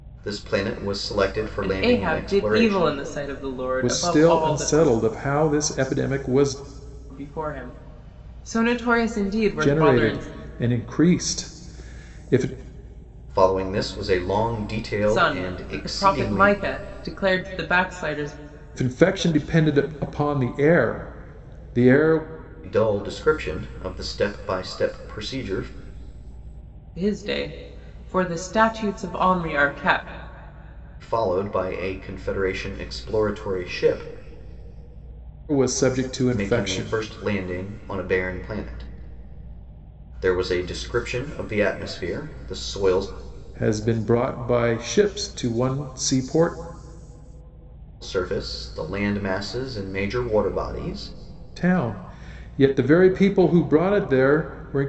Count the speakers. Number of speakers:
three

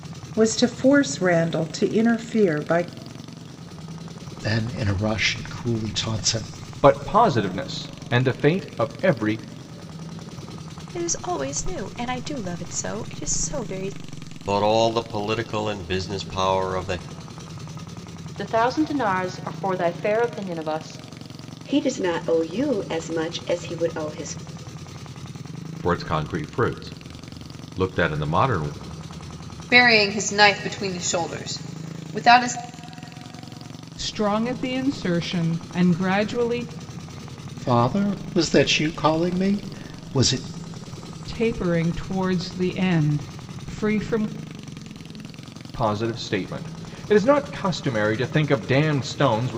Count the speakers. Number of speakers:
ten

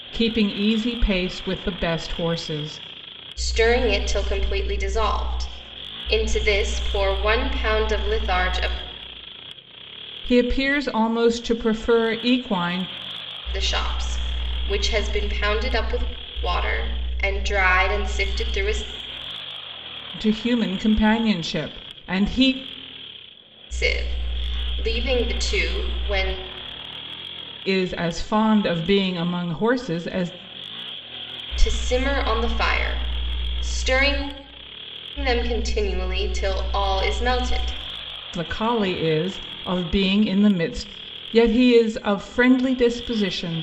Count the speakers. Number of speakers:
two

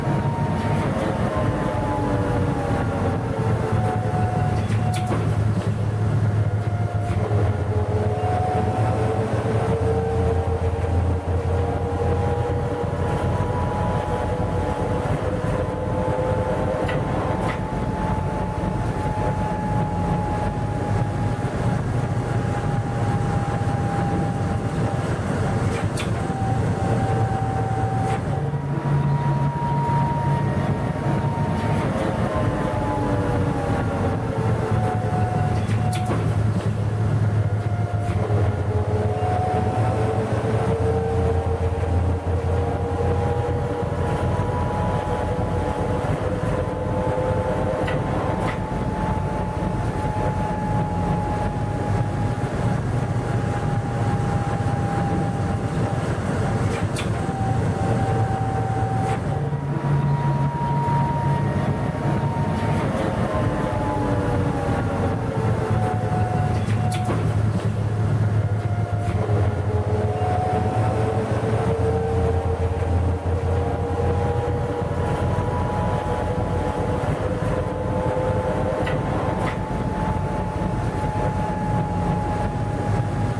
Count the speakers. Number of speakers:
zero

